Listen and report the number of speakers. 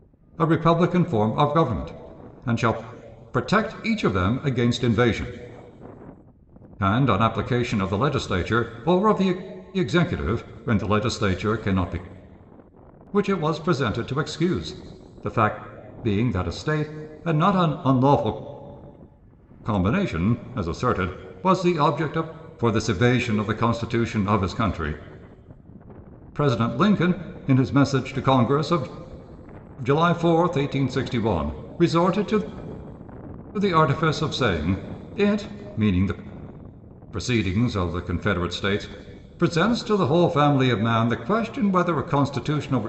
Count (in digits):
1